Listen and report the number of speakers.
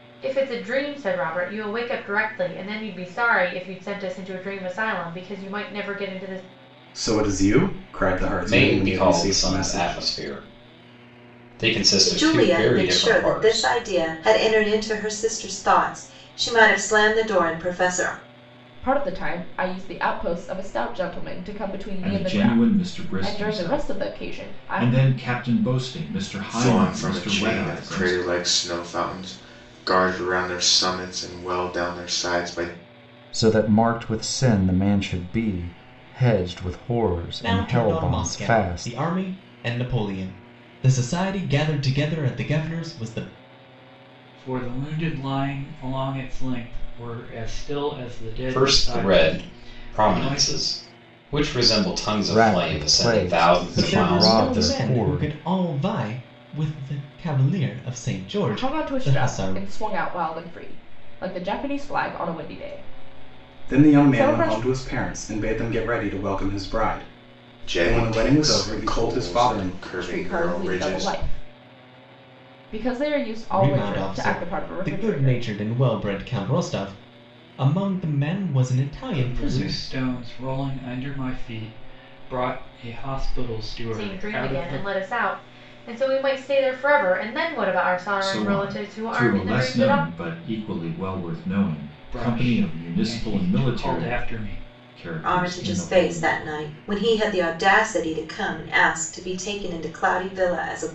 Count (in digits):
10